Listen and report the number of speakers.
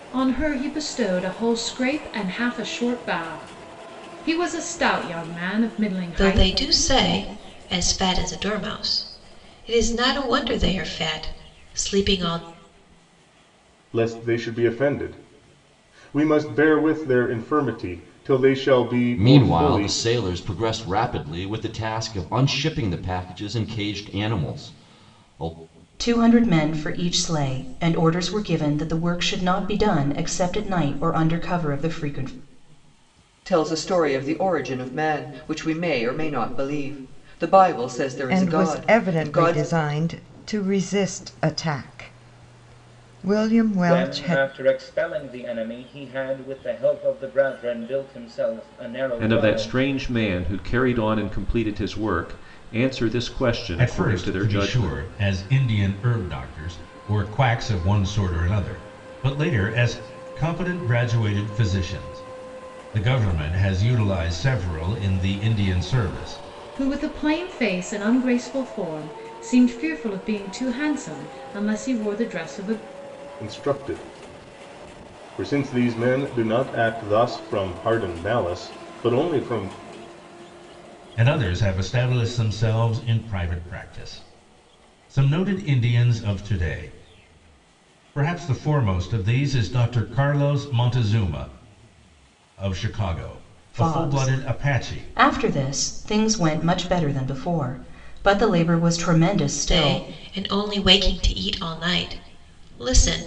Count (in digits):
10